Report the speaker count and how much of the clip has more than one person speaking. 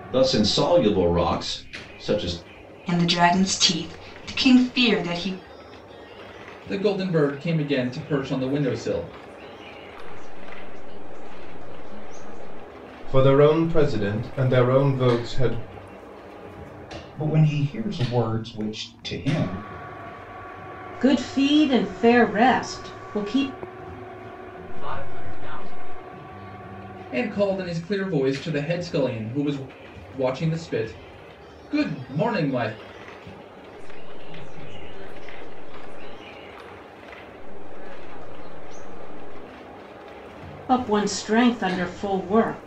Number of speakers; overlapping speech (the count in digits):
8, no overlap